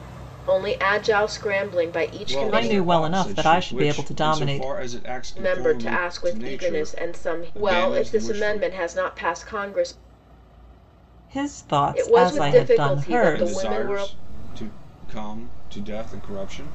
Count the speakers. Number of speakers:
three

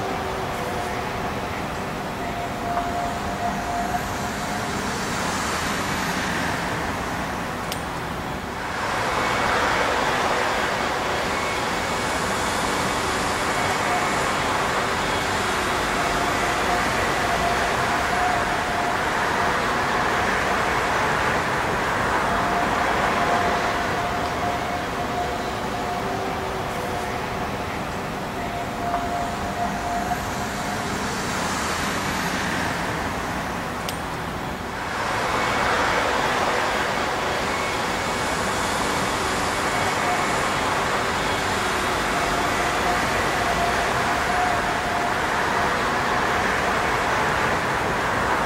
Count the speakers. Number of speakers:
zero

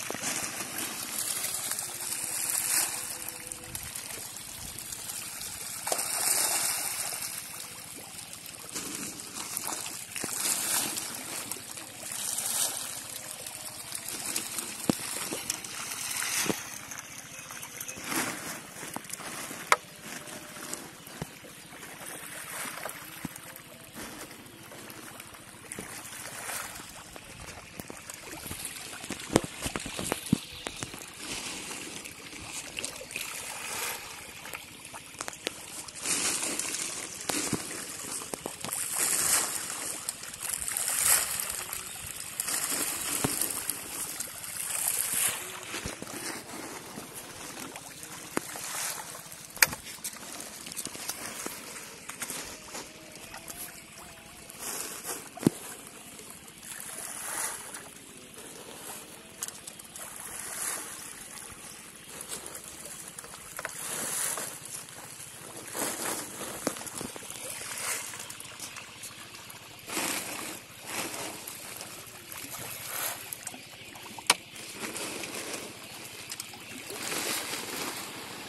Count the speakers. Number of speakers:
zero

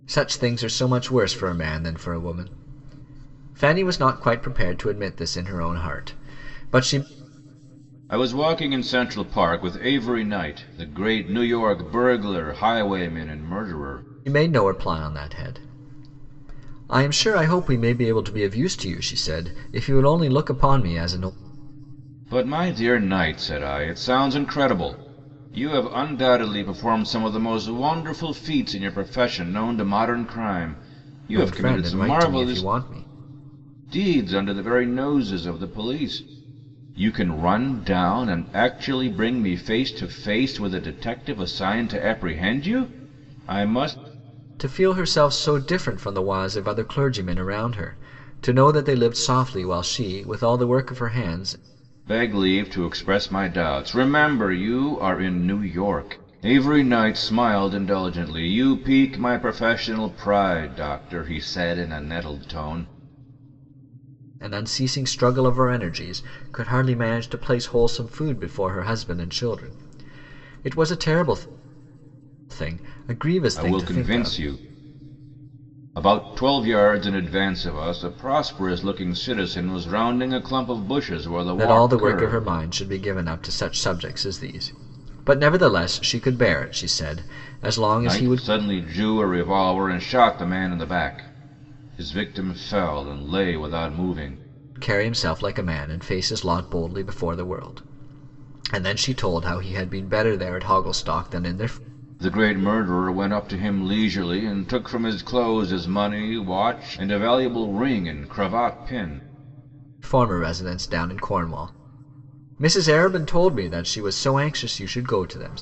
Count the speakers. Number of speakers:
two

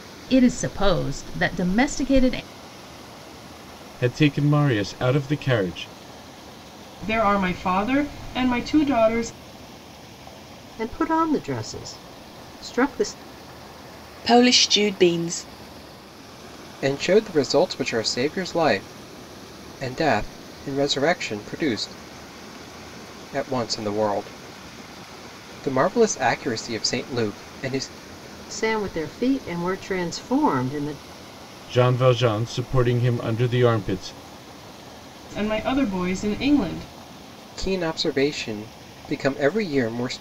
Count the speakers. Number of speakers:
six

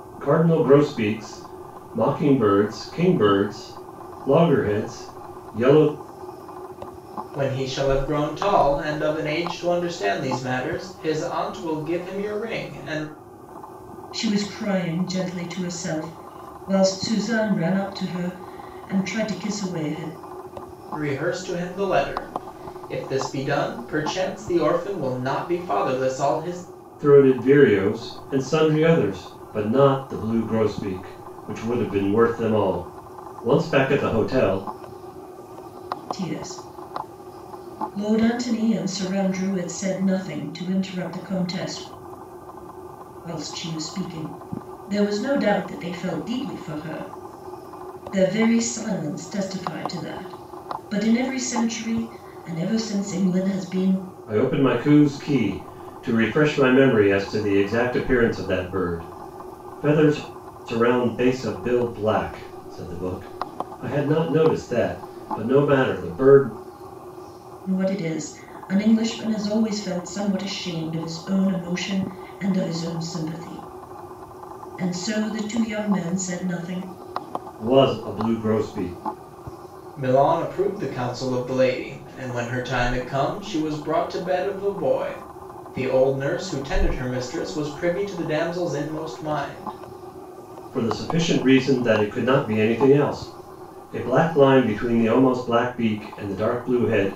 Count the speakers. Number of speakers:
three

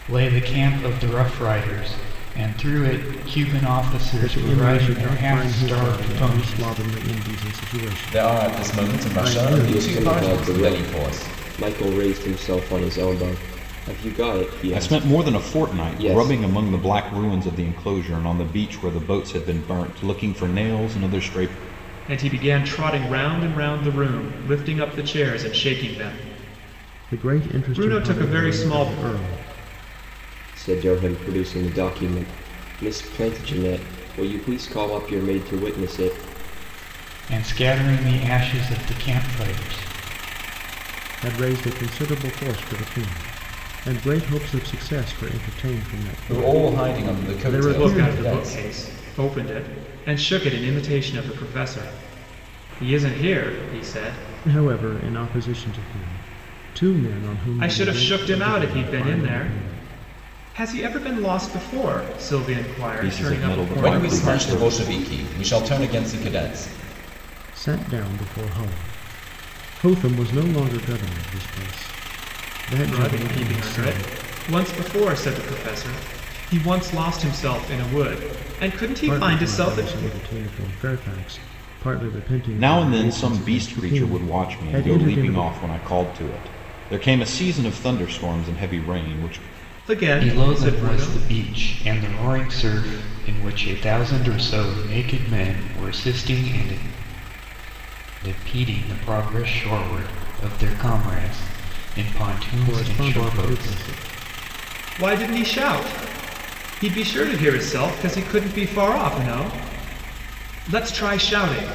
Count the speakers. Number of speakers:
six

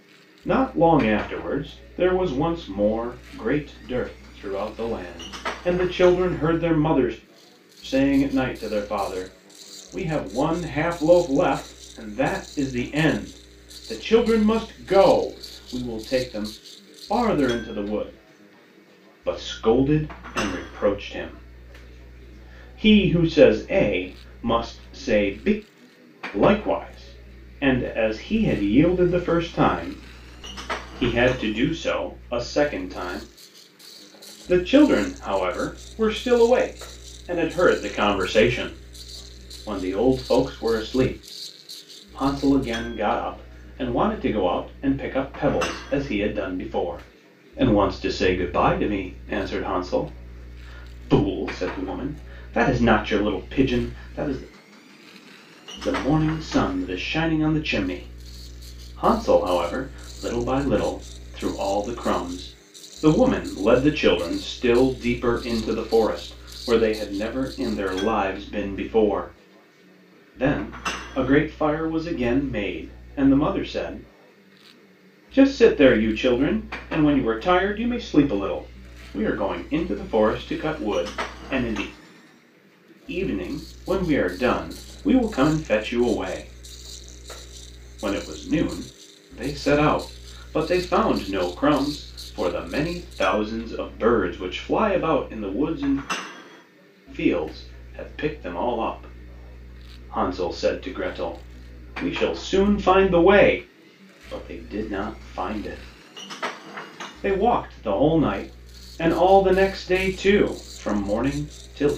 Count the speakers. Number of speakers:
one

